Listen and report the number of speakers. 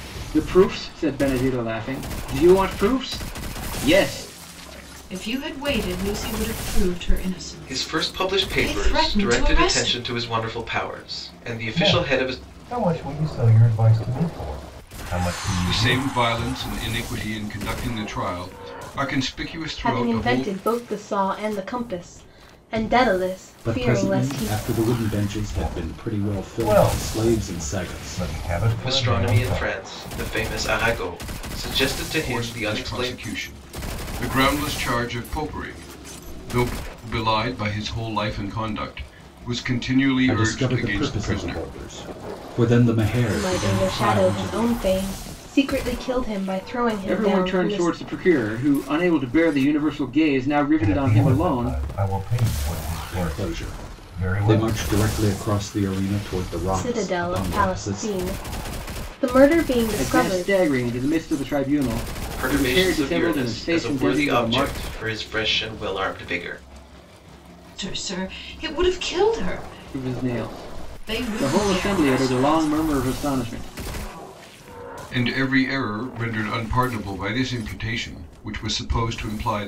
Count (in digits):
7